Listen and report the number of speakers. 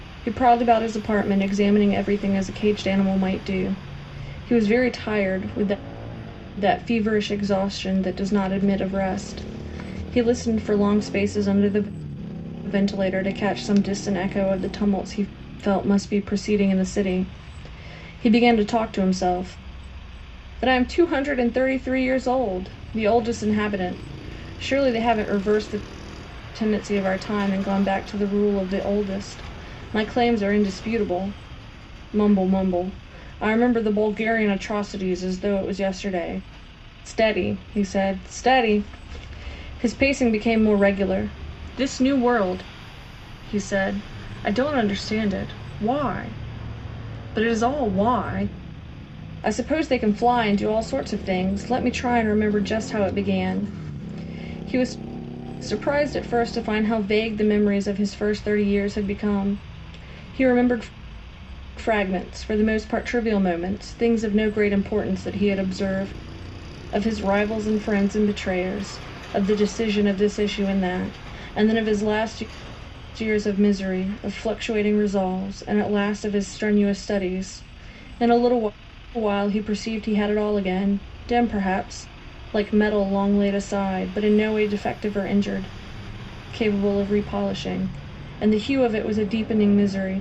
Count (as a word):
one